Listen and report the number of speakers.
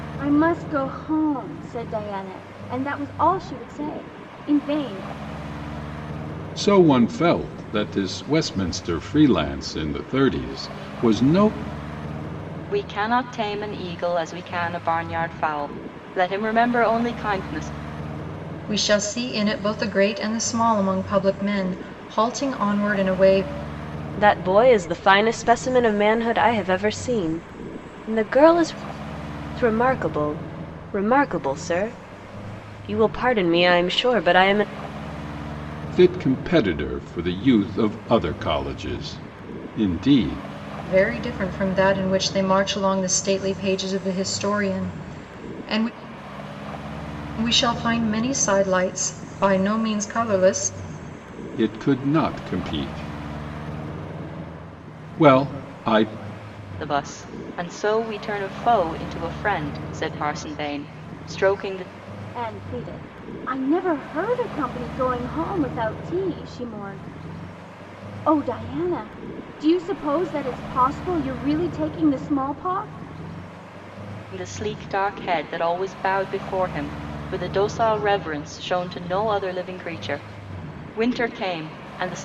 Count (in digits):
5